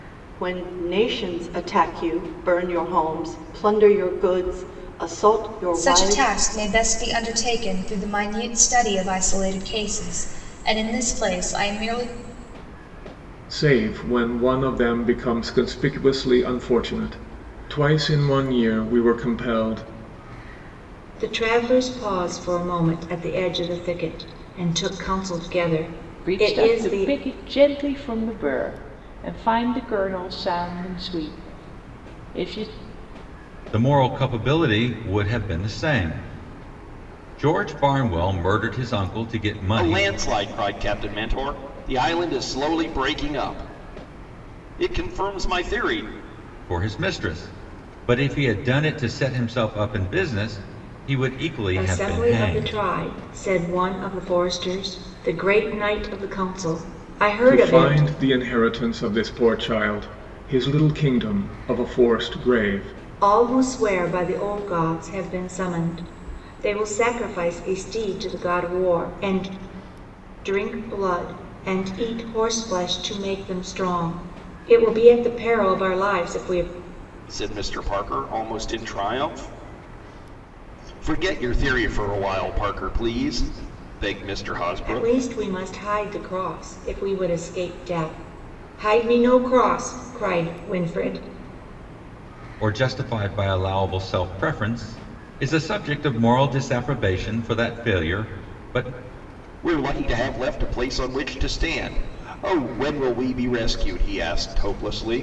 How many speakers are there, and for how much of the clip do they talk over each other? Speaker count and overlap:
seven, about 4%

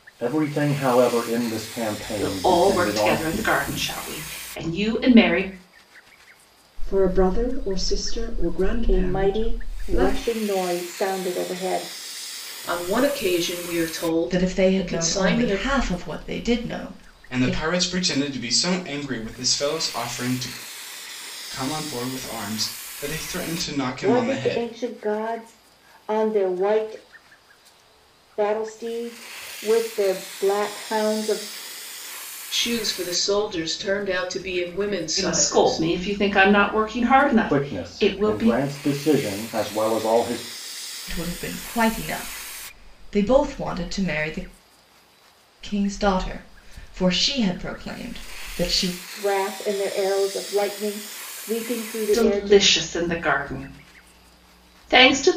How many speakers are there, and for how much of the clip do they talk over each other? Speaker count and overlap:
seven, about 14%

